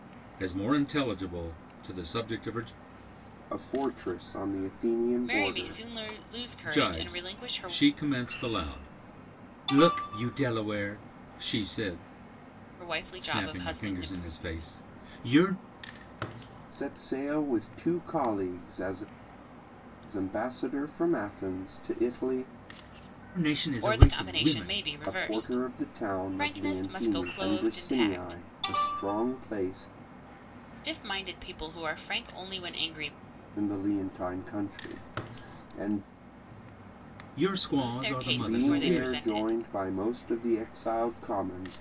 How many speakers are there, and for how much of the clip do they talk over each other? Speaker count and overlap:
3, about 21%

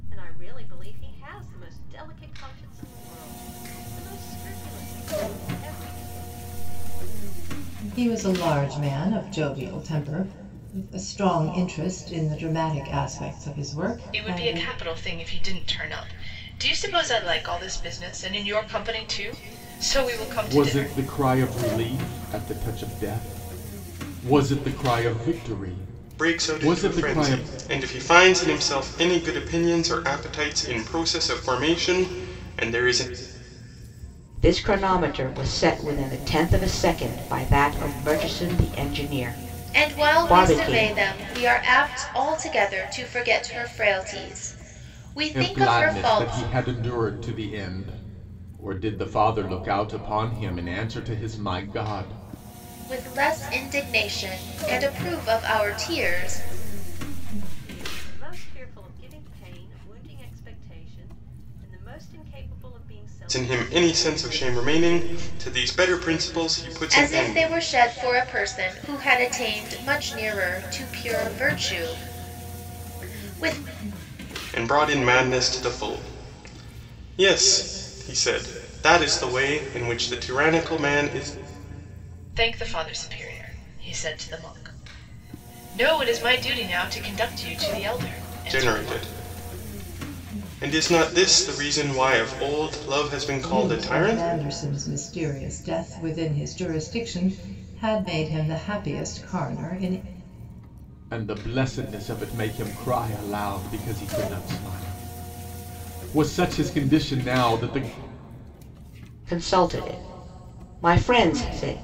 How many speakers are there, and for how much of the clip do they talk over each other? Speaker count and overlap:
7, about 8%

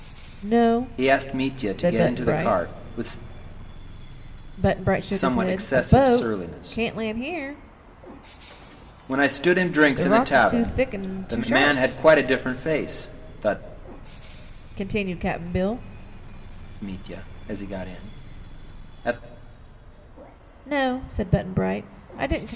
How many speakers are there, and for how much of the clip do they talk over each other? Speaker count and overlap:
2, about 24%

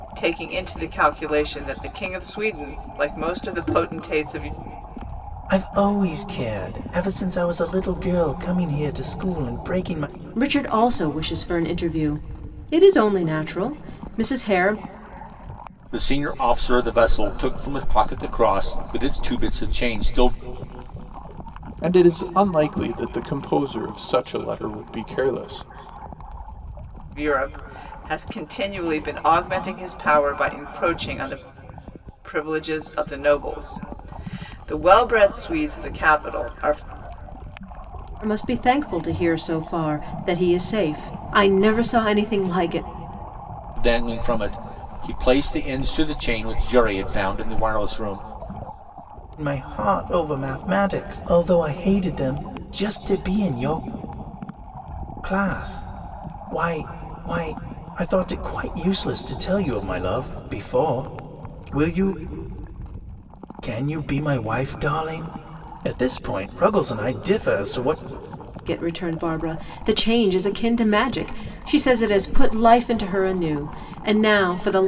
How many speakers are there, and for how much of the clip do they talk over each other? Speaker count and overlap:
5, no overlap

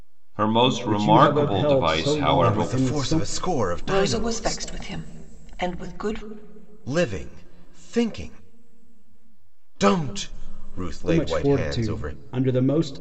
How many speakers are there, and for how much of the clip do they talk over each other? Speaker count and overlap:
4, about 33%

